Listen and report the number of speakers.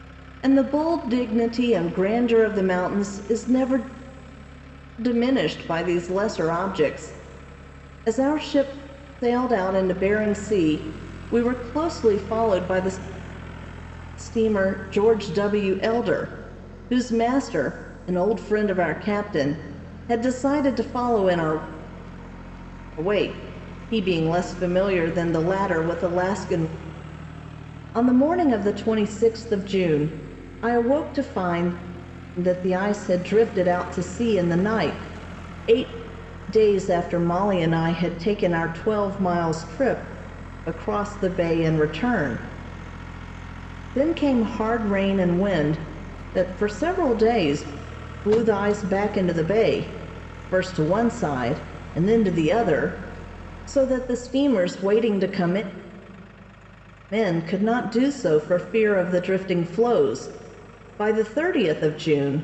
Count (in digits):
1